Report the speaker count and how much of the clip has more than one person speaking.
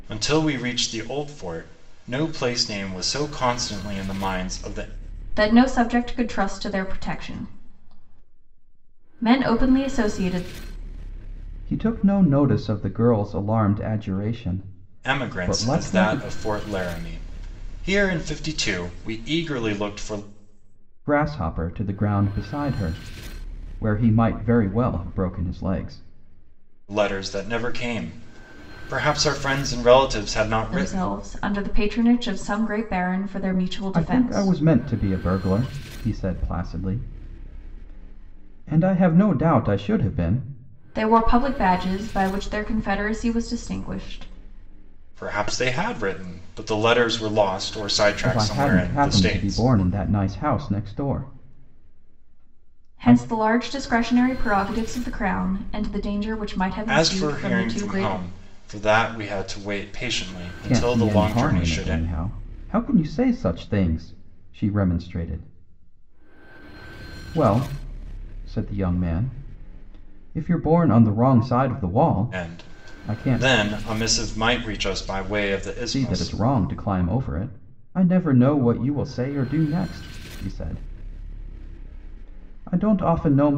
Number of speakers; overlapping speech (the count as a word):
three, about 10%